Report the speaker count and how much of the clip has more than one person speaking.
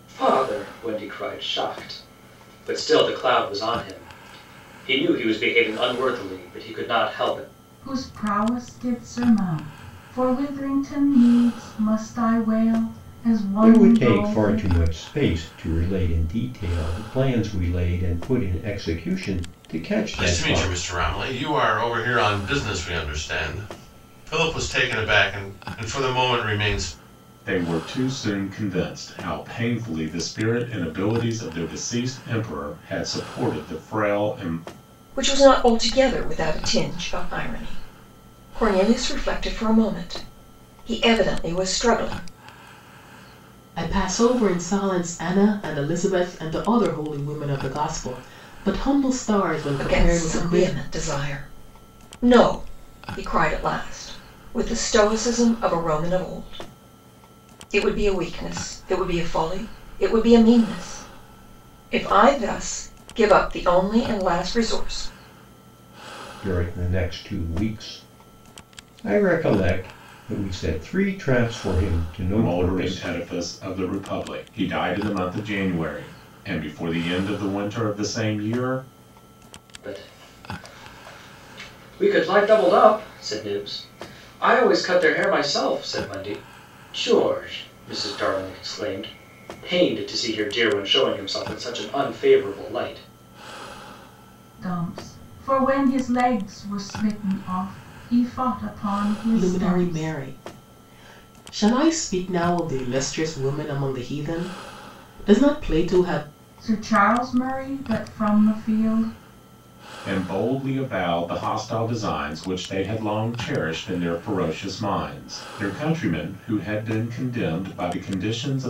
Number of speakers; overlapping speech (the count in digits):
7, about 4%